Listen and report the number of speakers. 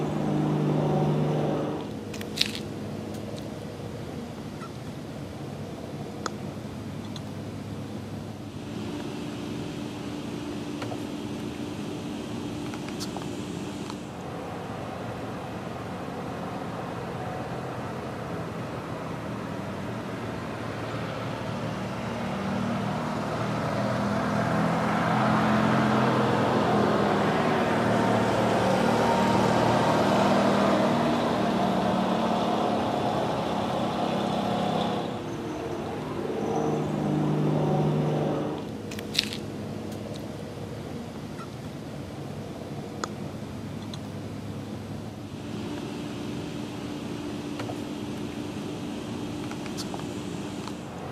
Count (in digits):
0